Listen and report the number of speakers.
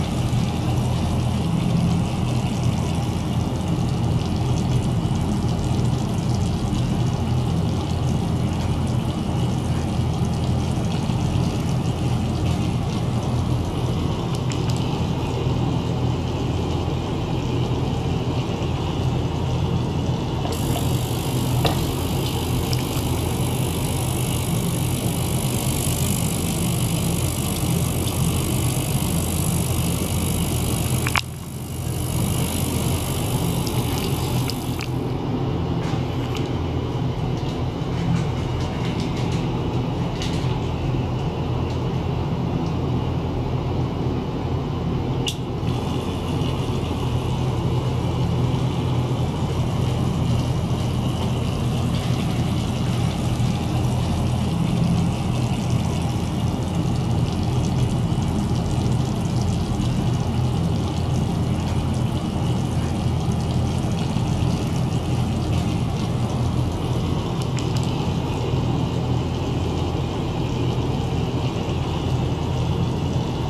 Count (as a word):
zero